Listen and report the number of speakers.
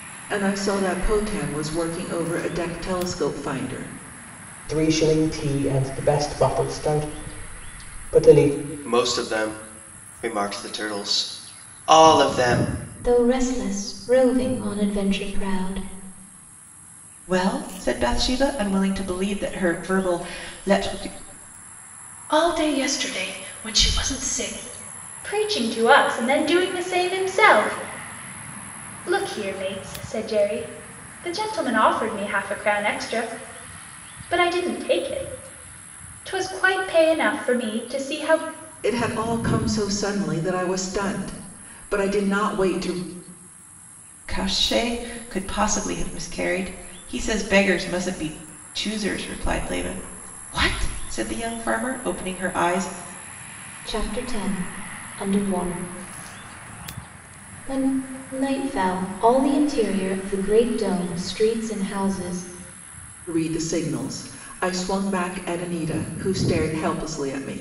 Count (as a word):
seven